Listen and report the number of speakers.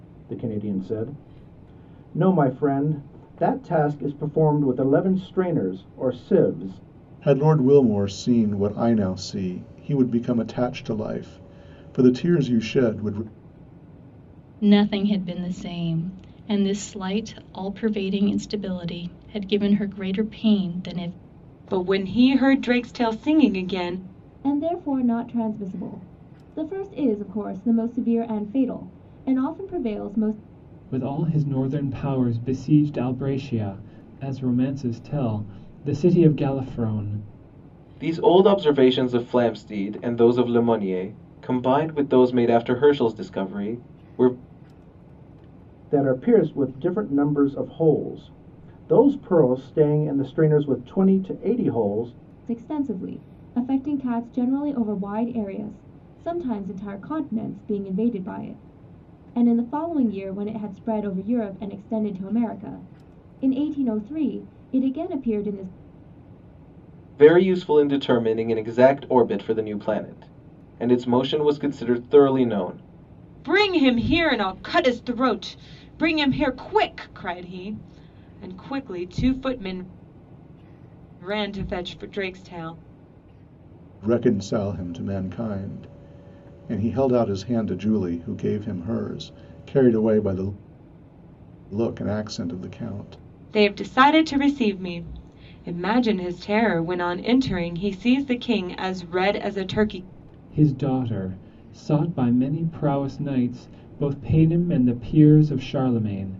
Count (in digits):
7